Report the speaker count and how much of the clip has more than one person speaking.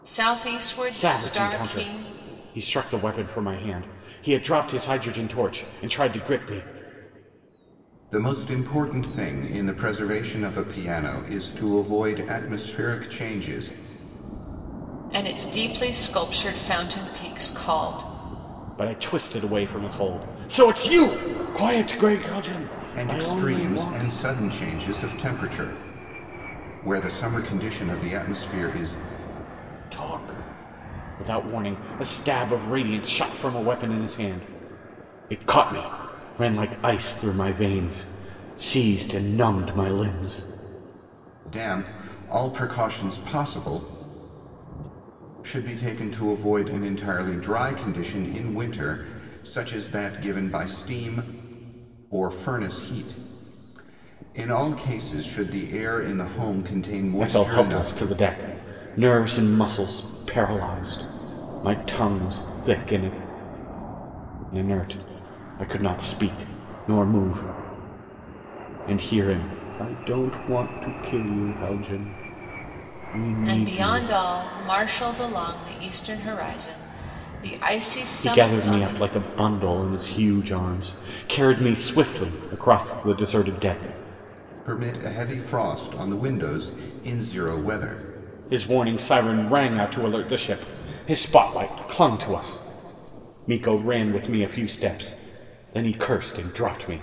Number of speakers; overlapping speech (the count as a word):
three, about 5%